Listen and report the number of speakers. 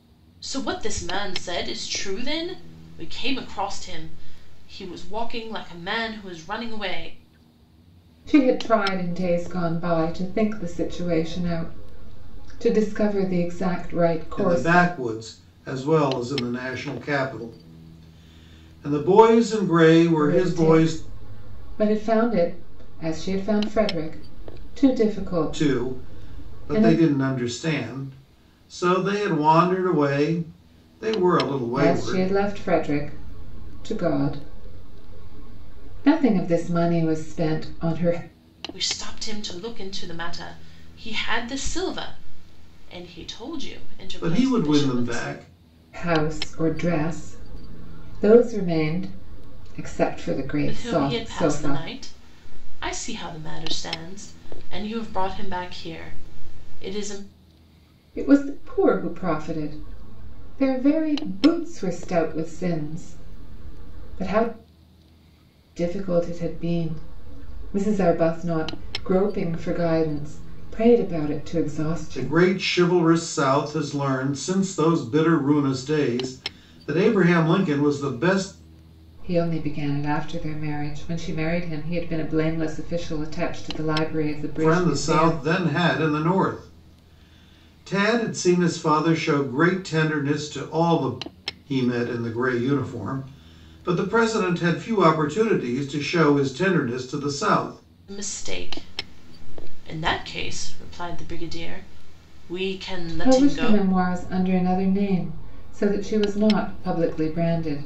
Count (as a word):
three